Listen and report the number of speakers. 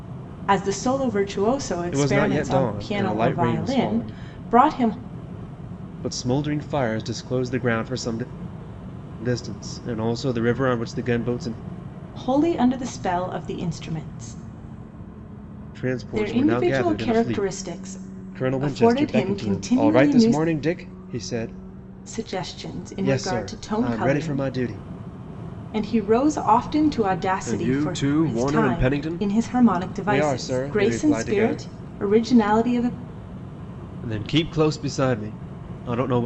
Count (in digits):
2